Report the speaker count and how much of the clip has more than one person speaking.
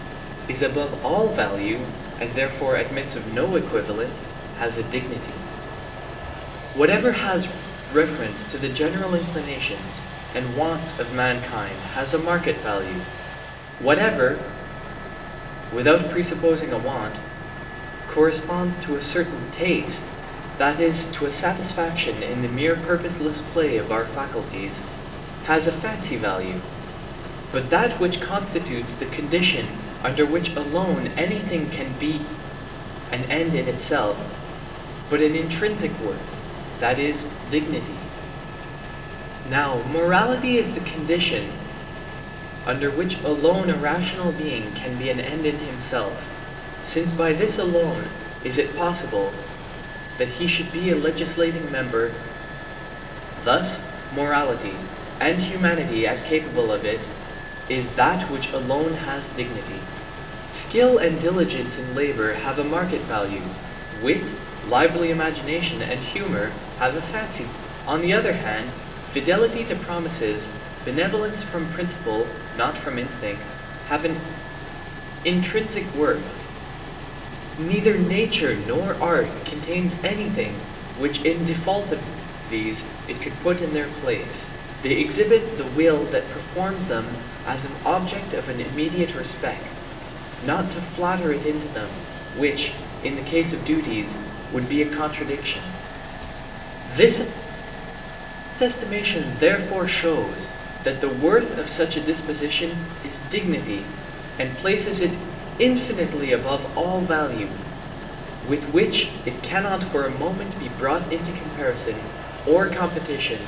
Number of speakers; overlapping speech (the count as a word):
one, no overlap